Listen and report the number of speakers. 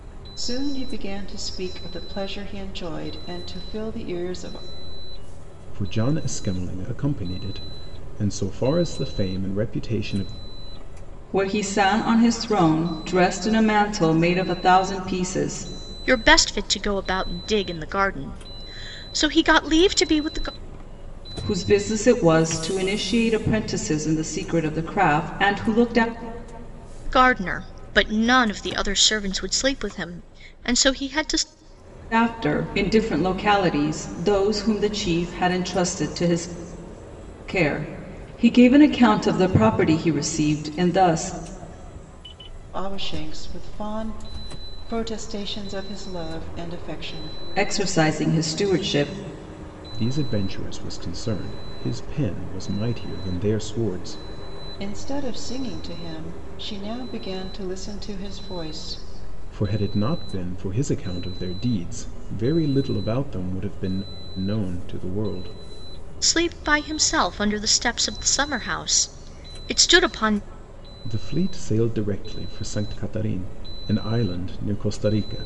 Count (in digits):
4